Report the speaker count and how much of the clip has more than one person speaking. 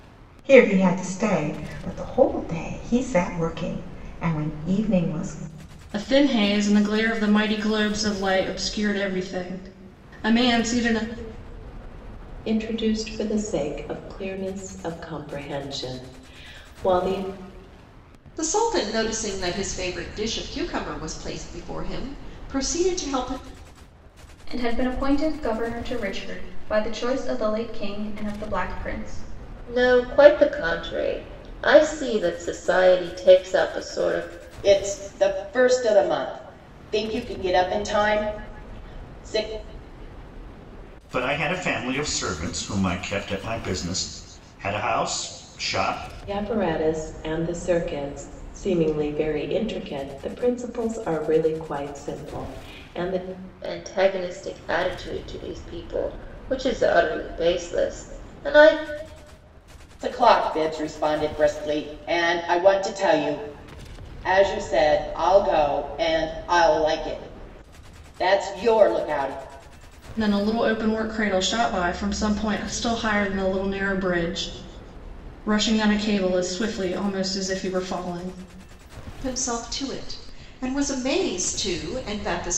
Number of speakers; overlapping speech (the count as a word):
eight, no overlap